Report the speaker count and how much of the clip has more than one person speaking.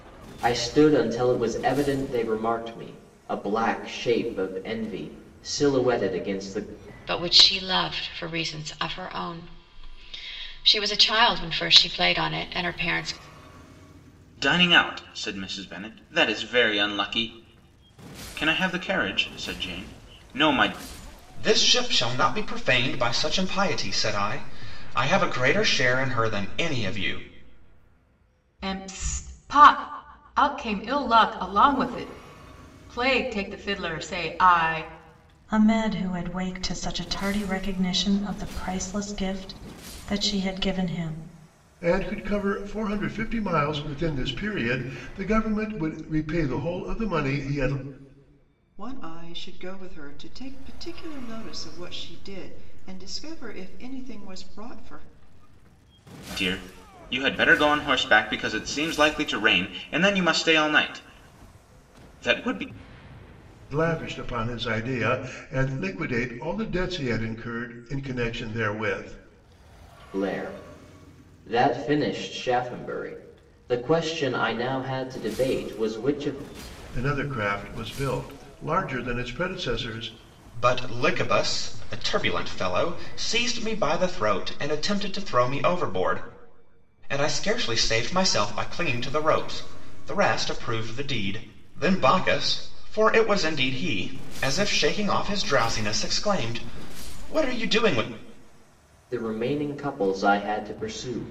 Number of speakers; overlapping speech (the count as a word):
eight, no overlap